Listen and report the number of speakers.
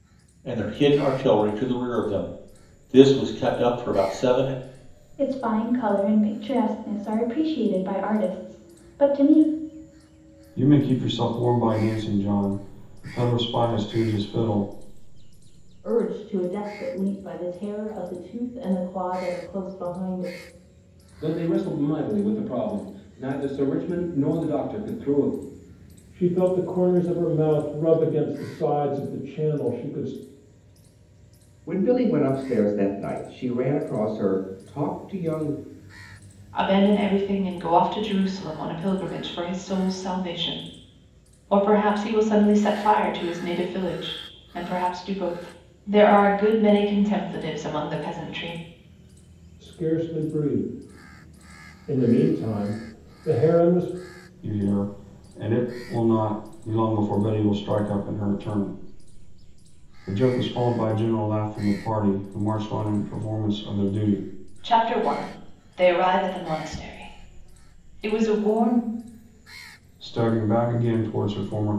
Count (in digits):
8